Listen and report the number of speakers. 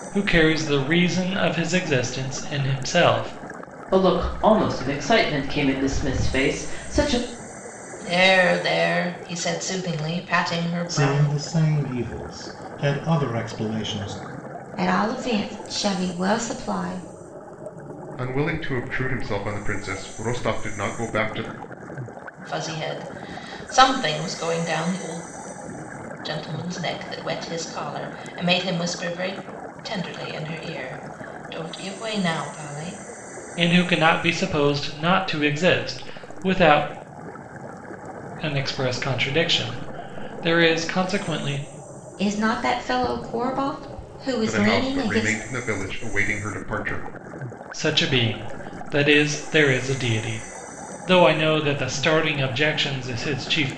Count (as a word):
six